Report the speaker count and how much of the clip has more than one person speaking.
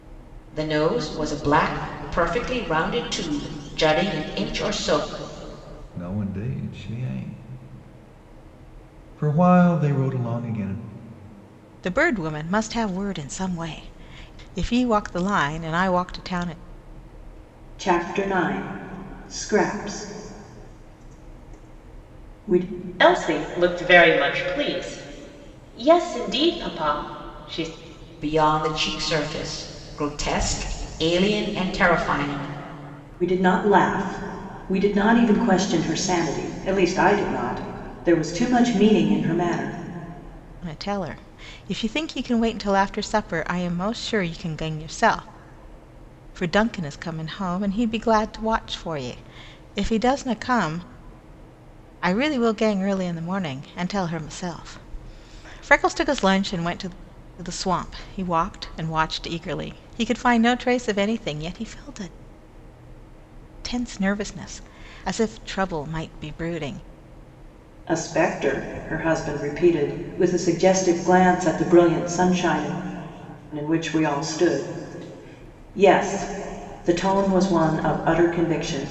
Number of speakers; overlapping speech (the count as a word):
five, no overlap